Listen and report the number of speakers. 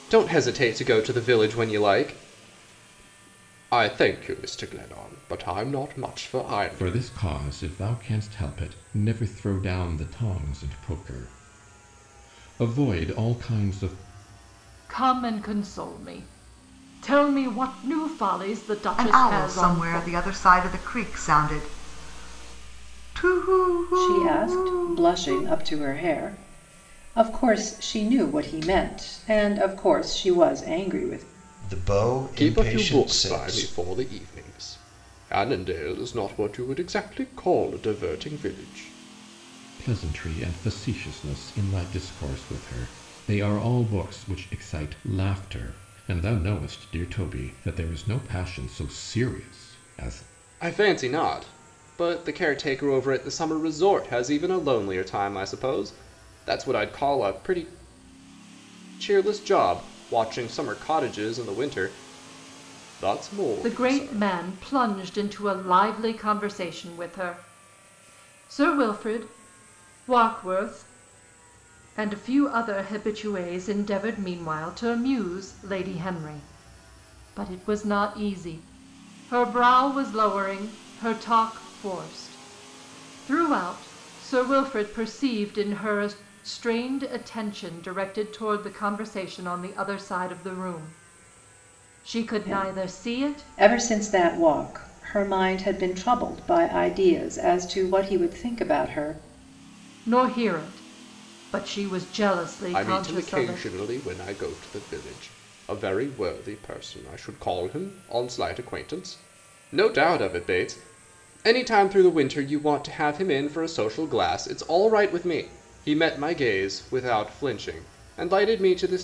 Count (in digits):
6